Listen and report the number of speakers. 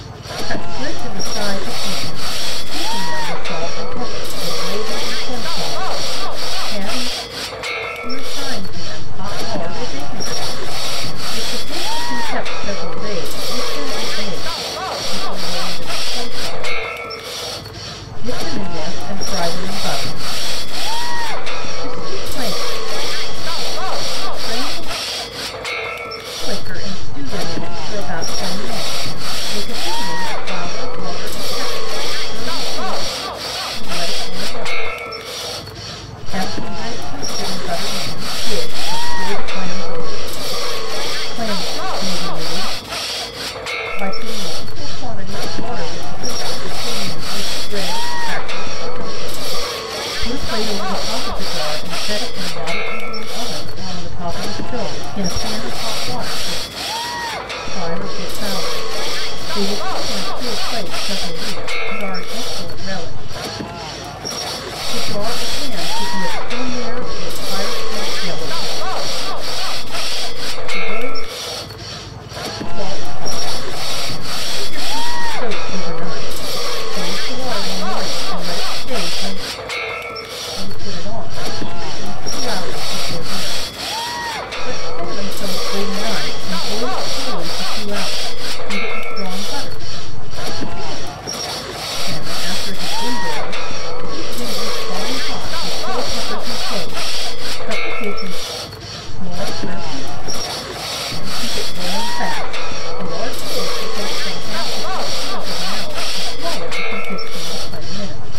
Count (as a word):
one